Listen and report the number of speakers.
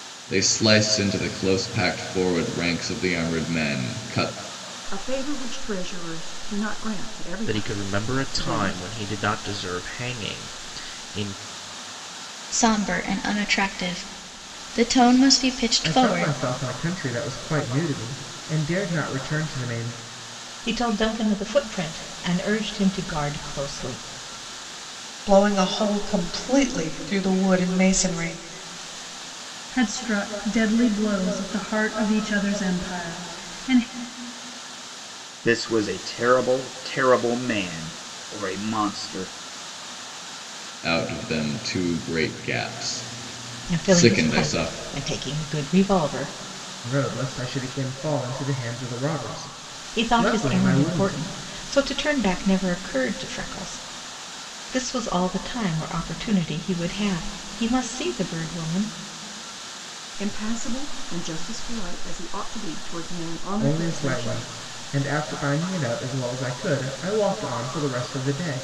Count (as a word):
nine